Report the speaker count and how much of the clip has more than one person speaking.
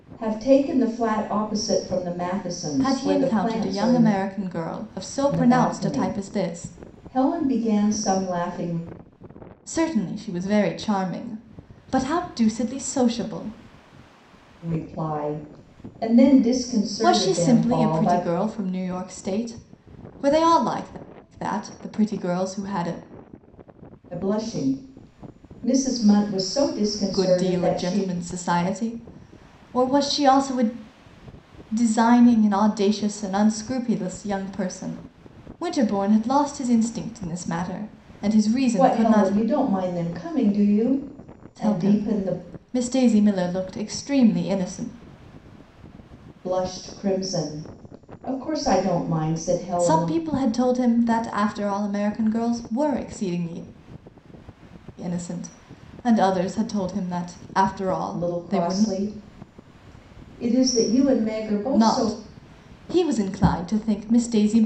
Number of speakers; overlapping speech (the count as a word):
two, about 13%